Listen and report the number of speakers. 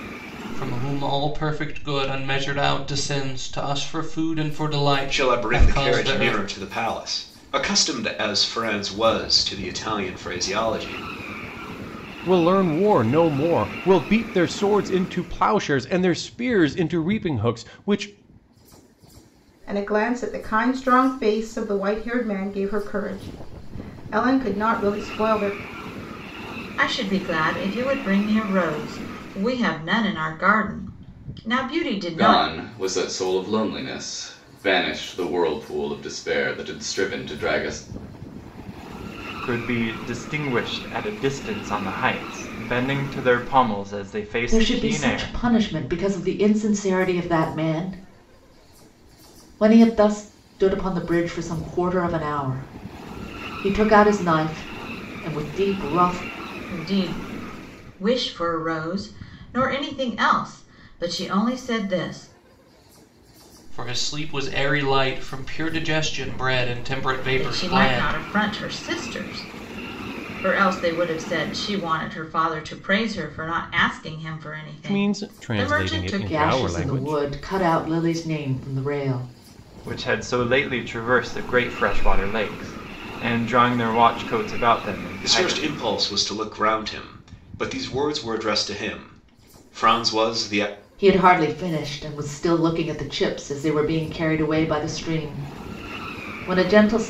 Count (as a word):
eight